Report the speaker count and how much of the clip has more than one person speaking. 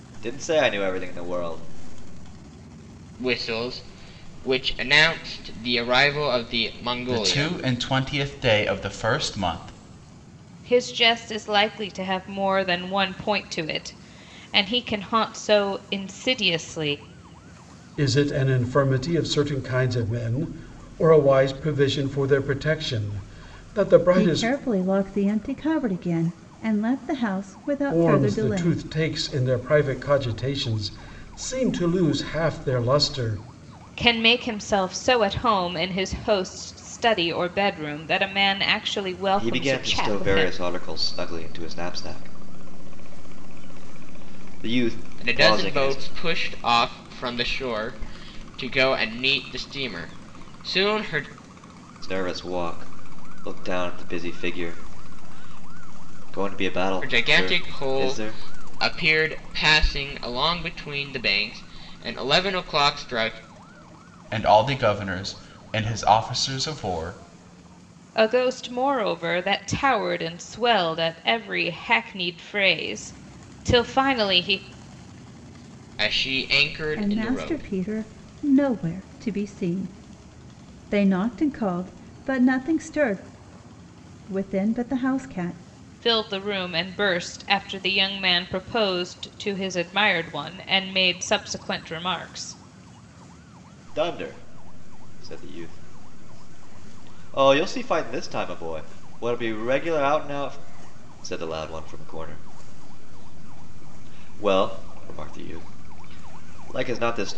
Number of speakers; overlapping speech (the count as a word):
six, about 6%